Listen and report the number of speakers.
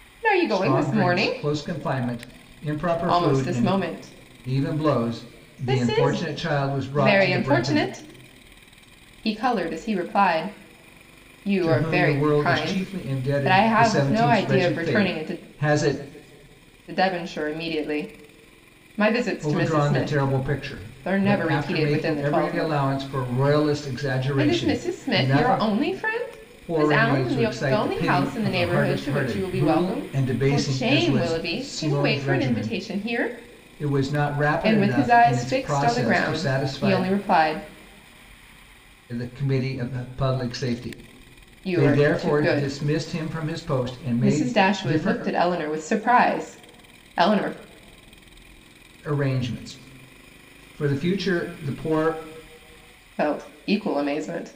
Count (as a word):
two